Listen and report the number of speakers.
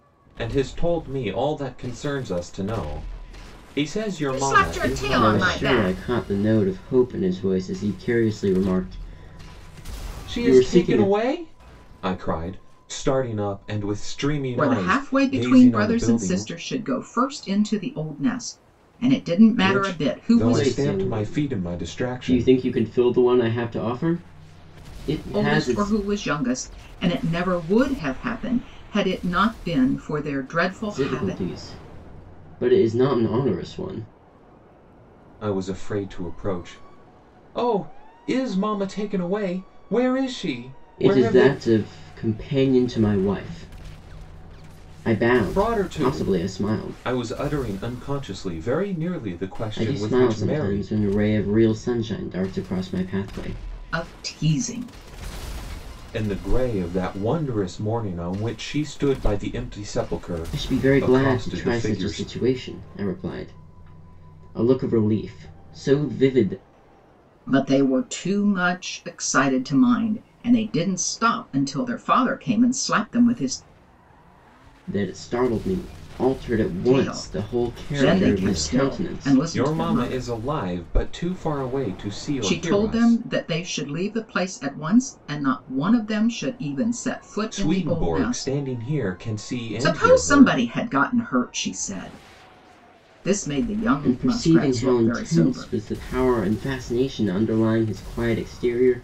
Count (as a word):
three